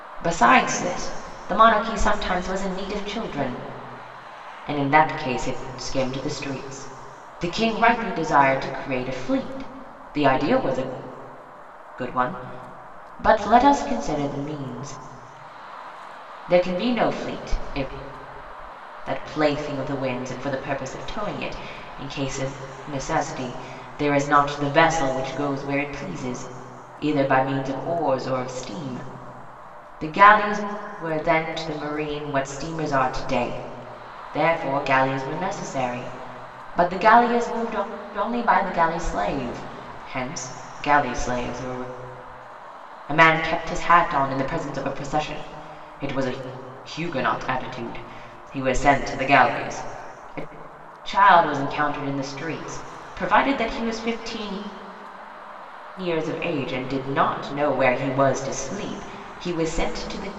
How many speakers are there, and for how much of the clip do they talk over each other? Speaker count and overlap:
1, no overlap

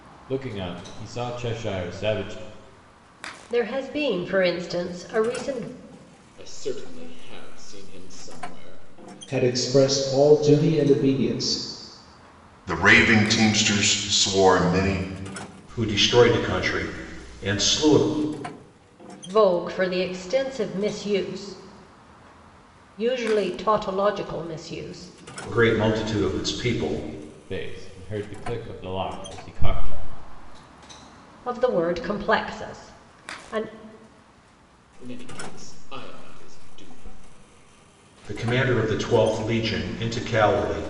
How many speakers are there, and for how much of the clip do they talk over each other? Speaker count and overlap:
6, no overlap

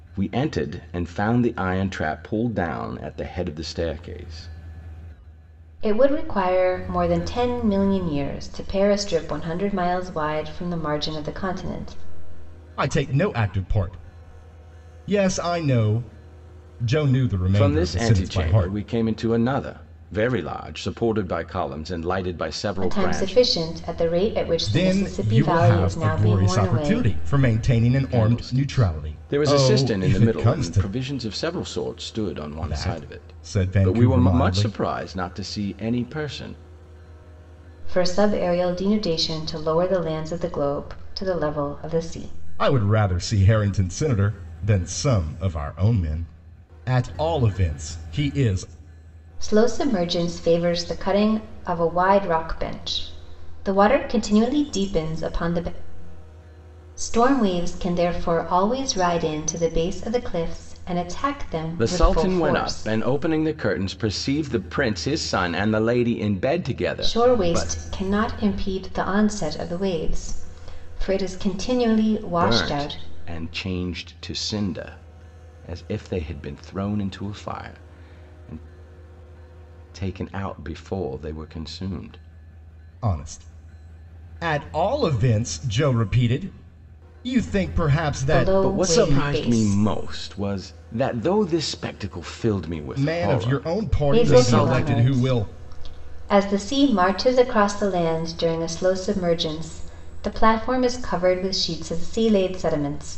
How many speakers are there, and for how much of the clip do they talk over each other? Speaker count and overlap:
3, about 16%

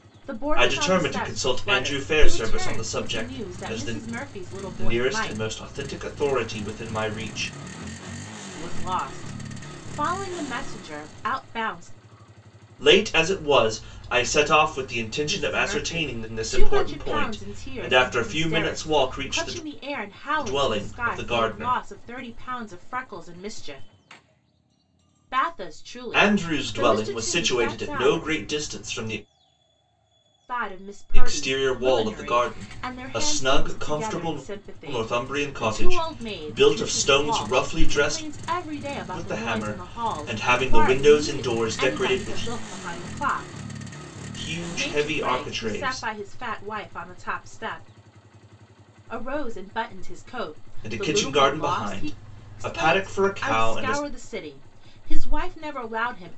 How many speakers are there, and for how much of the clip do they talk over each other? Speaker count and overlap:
2, about 47%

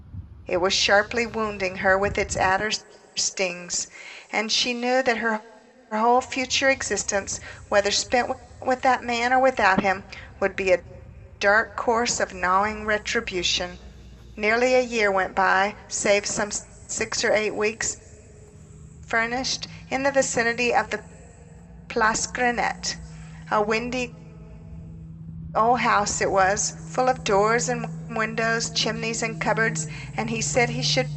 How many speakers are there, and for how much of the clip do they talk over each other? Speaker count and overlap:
1, no overlap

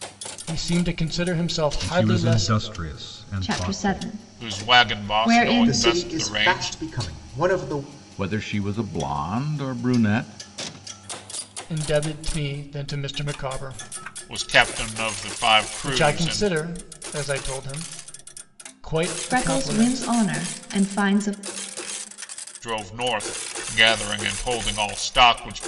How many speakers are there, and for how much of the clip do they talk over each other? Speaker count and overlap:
6, about 22%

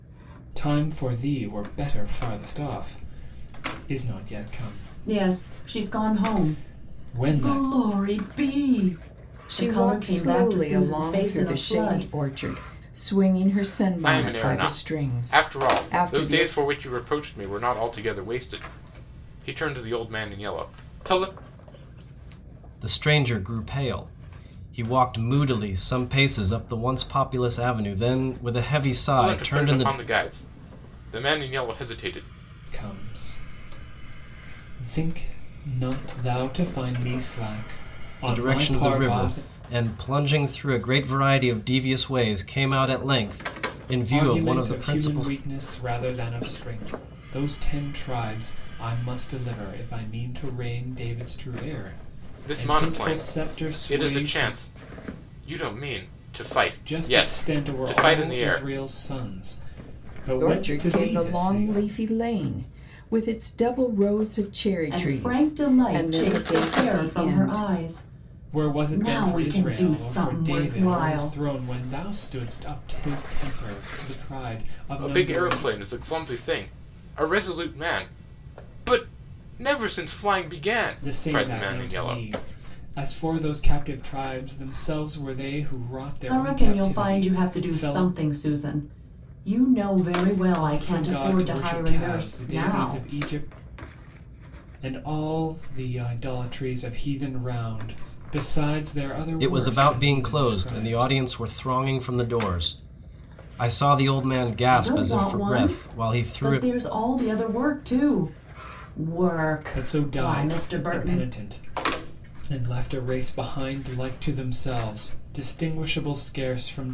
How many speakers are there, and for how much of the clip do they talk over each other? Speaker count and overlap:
5, about 29%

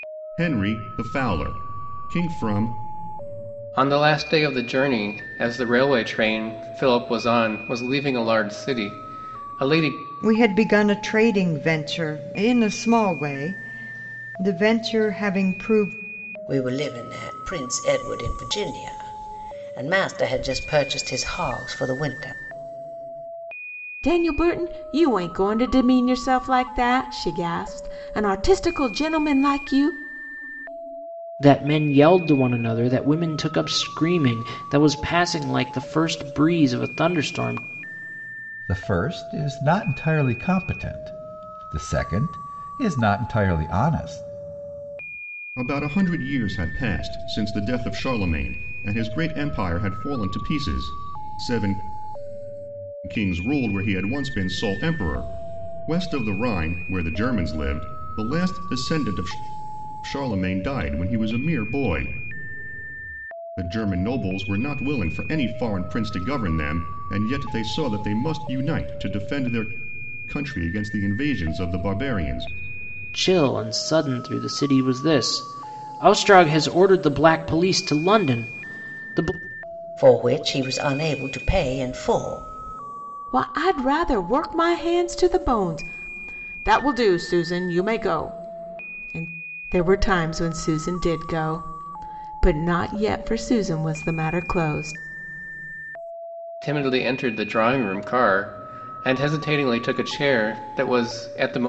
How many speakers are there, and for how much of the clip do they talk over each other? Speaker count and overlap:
7, no overlap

